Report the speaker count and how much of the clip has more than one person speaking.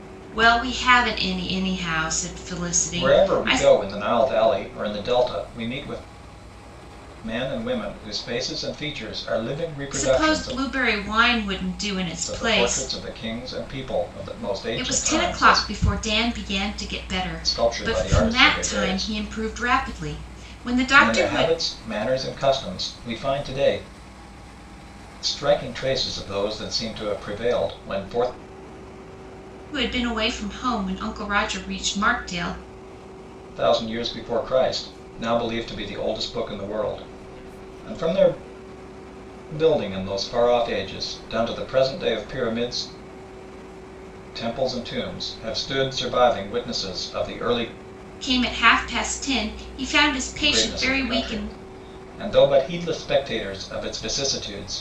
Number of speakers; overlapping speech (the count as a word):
two, about 12%